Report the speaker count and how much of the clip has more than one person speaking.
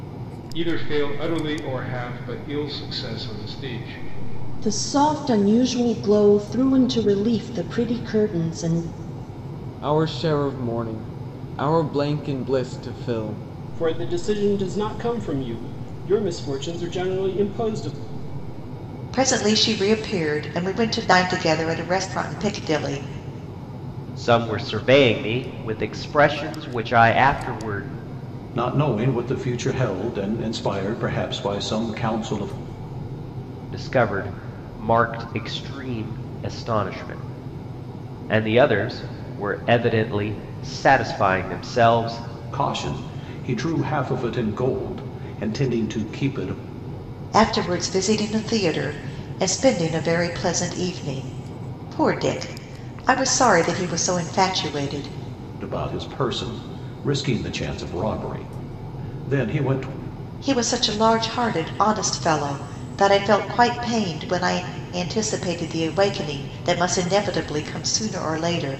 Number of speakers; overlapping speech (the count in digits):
7, no overlap